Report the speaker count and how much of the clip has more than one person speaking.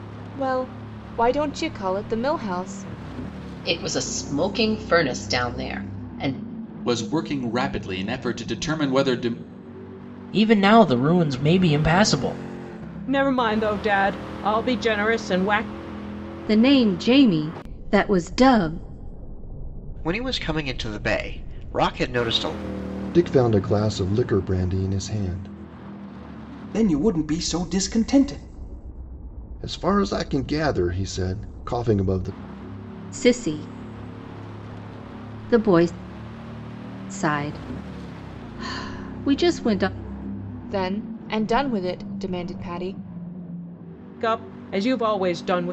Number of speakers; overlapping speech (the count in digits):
9, no overlap